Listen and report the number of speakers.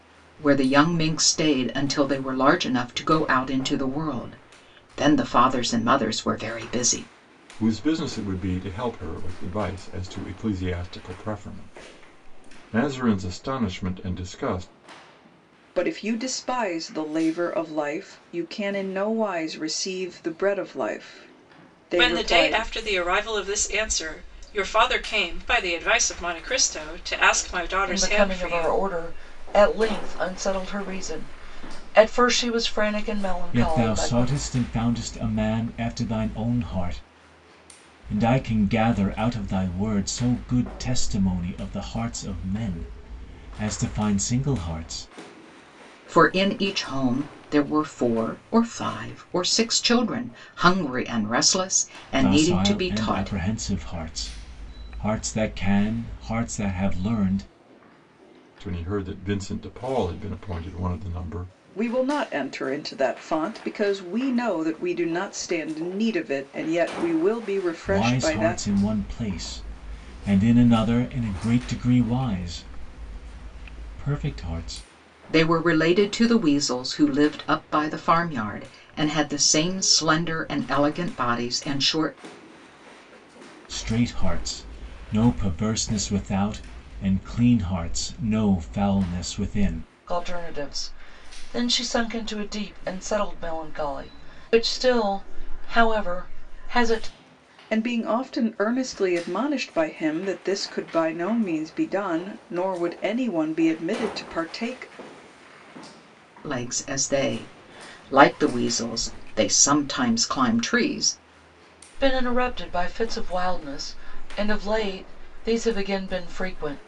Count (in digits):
6